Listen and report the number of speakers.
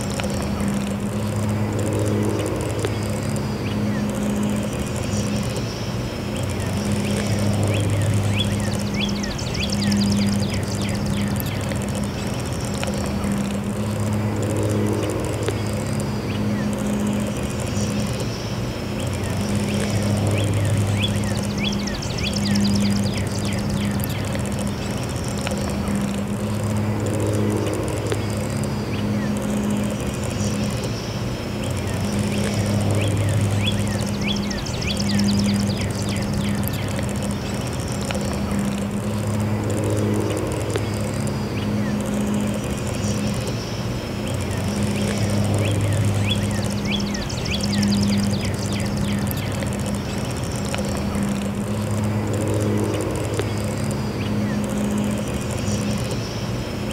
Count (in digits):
0